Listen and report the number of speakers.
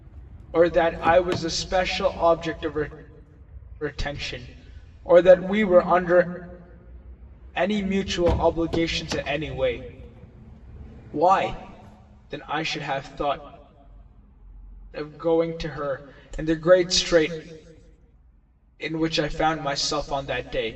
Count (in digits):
1